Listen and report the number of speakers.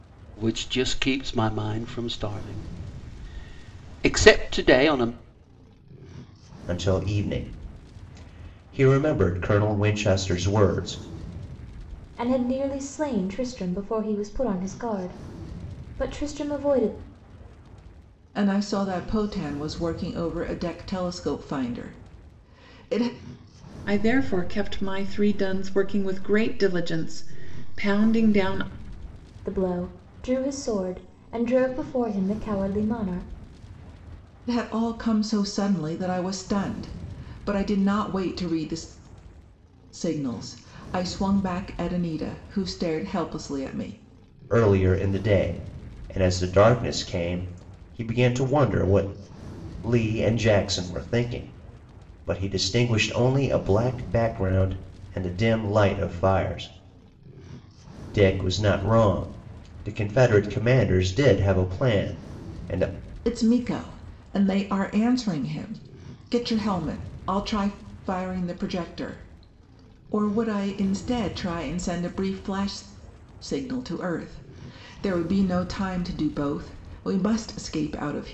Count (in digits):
5